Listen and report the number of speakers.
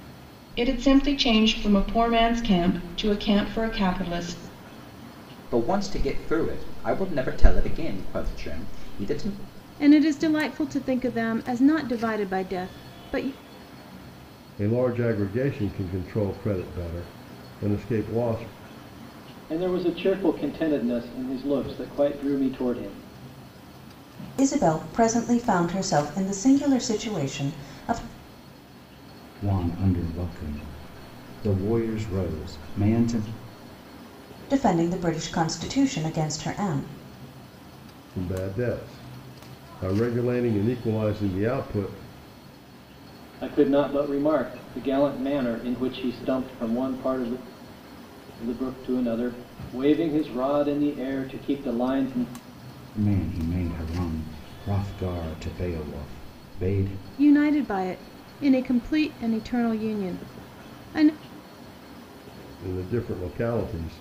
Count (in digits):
7